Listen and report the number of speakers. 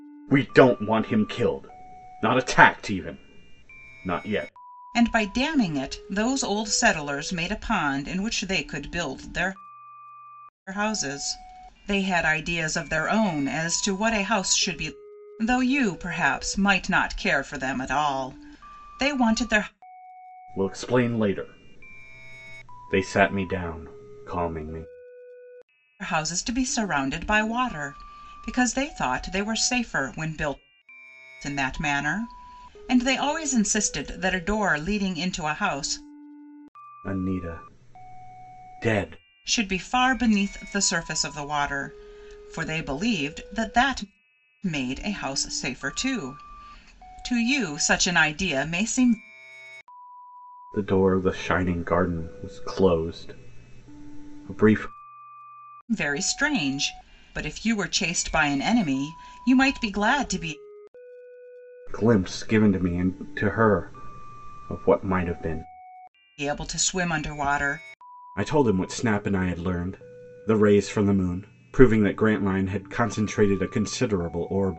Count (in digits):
2